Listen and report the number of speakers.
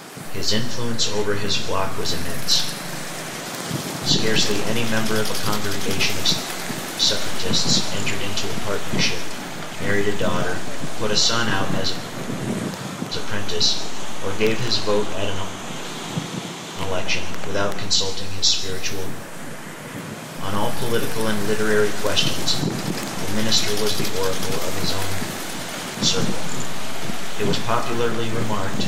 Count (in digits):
1